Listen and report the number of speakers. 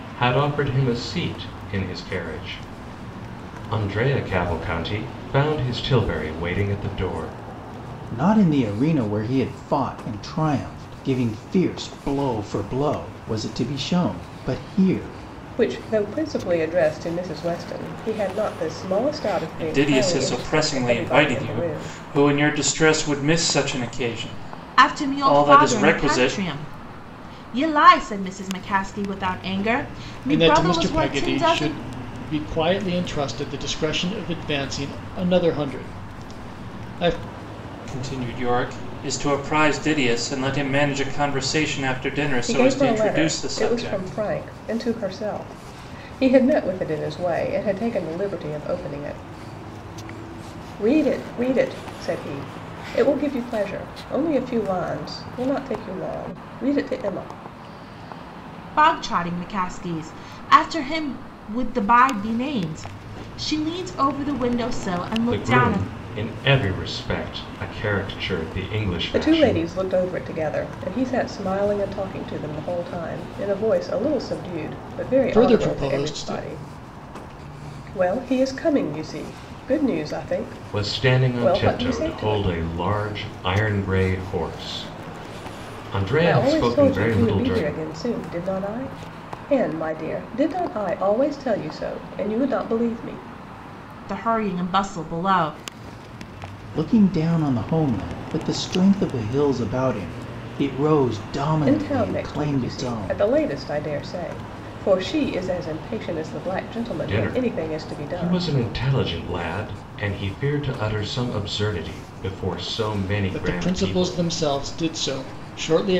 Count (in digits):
6